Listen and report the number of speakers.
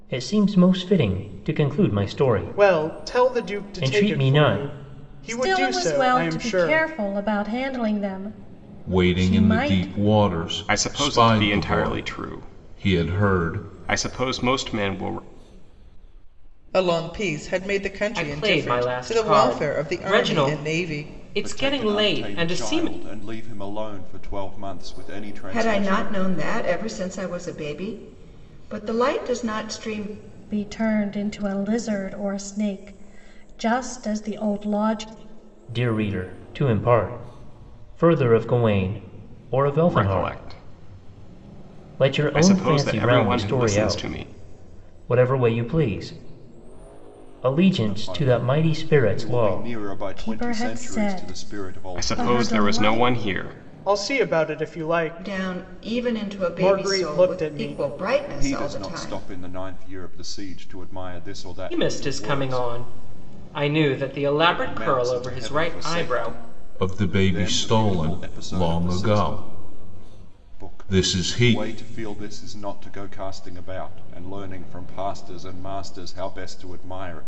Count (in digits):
9